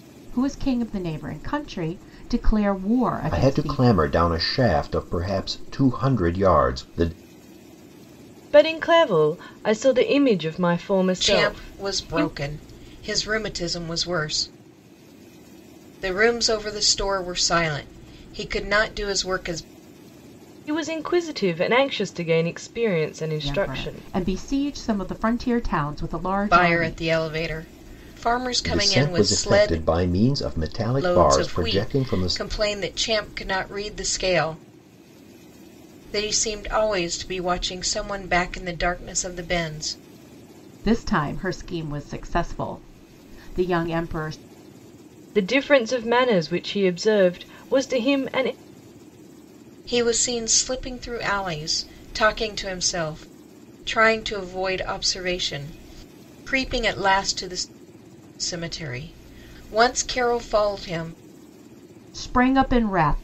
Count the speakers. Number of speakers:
4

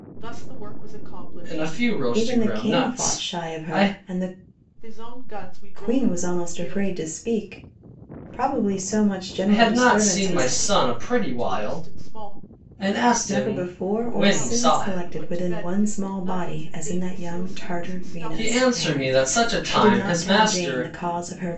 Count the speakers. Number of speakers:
3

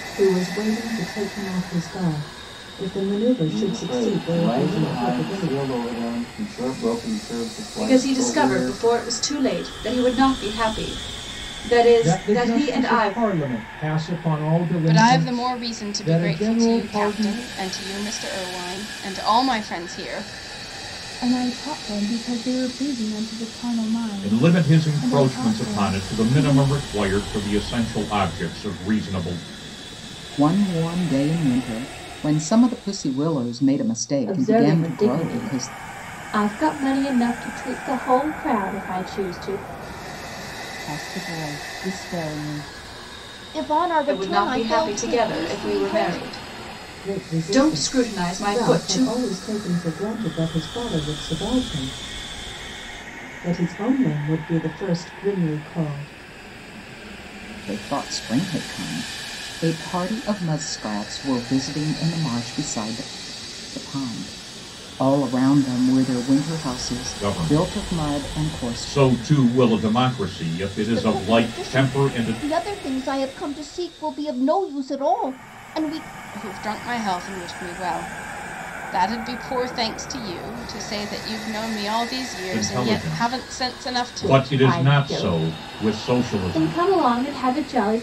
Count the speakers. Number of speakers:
10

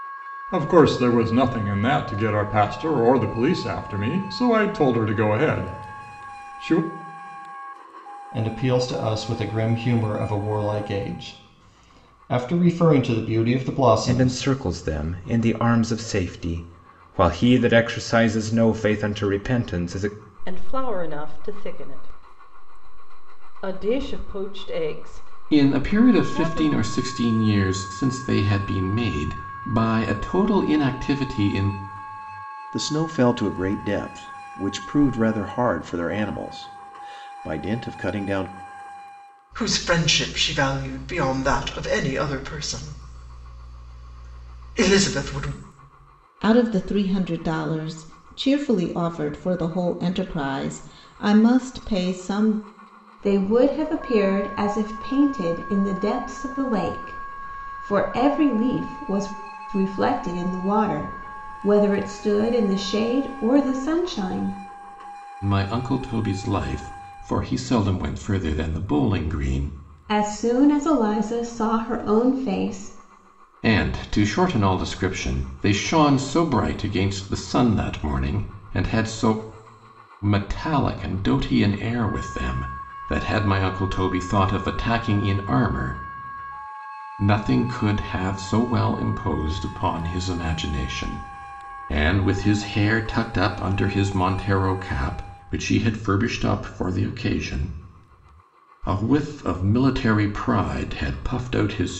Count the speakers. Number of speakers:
9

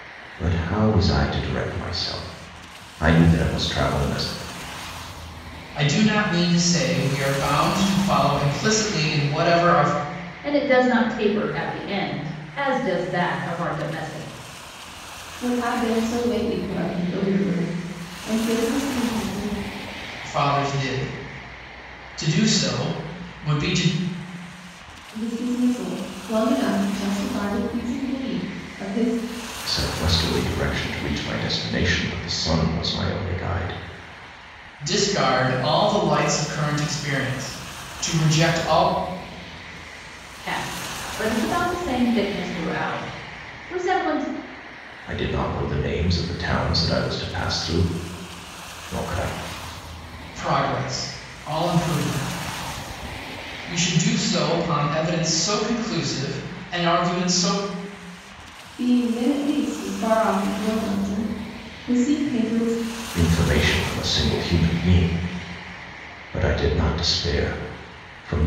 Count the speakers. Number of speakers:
4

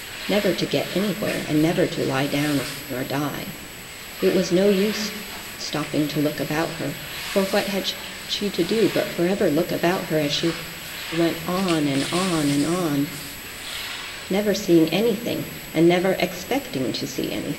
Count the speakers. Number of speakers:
1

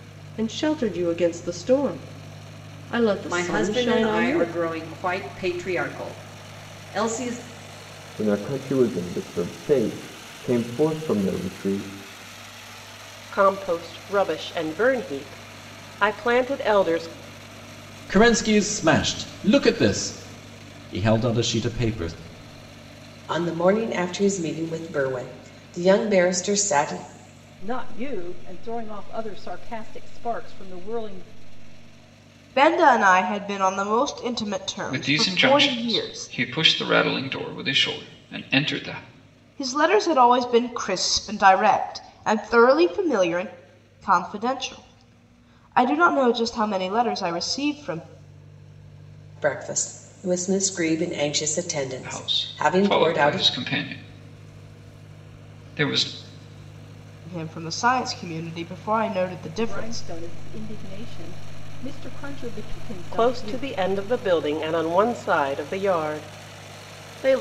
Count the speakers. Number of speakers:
9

